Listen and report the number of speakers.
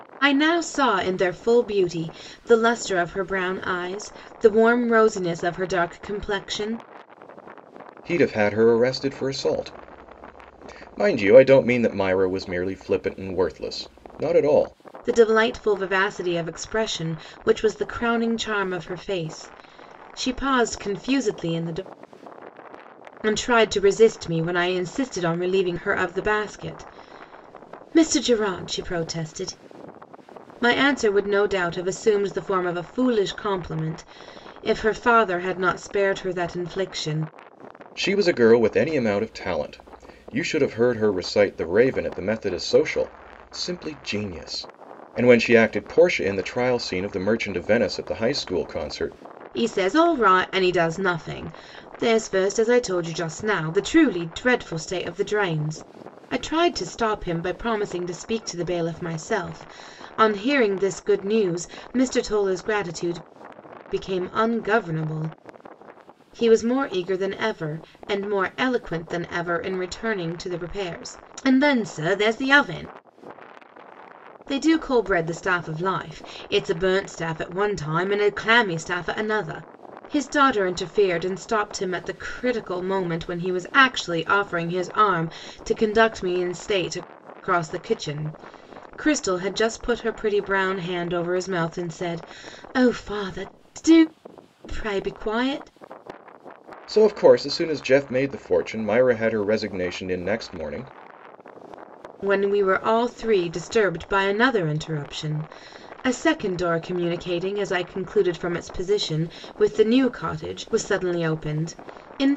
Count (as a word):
two